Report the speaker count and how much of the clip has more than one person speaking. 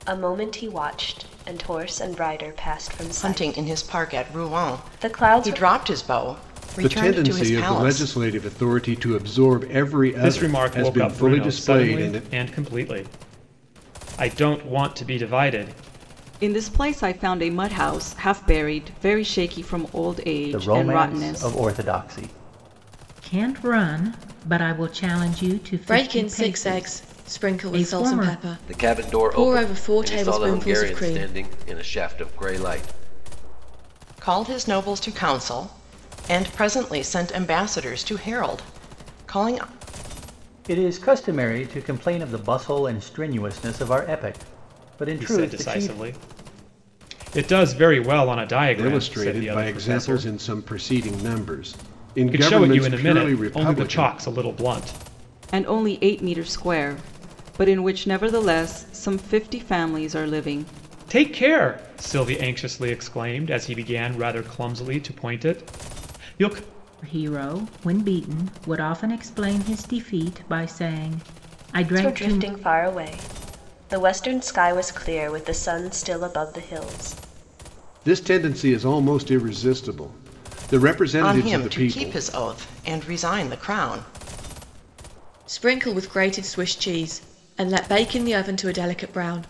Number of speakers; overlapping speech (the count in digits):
9, about 20%